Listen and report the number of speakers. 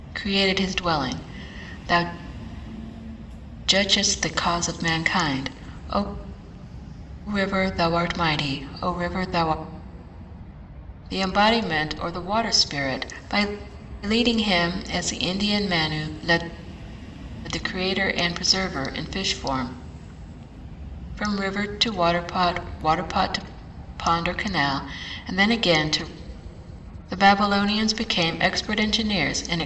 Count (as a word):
one